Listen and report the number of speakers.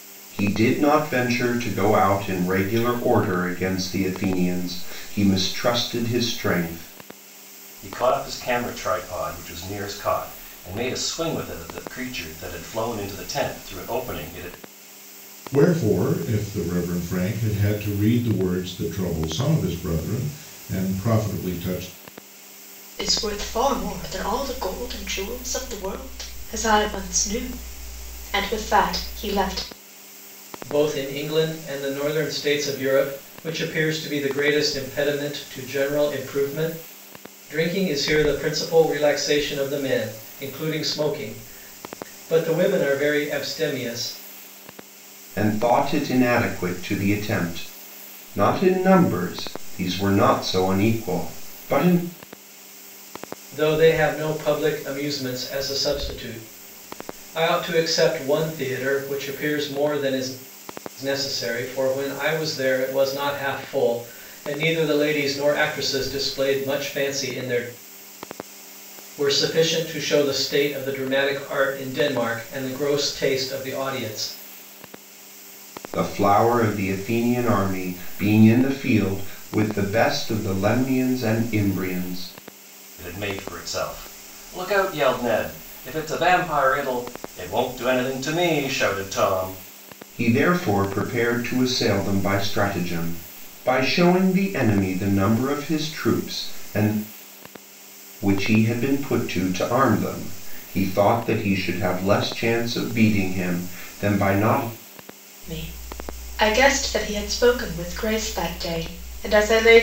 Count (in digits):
5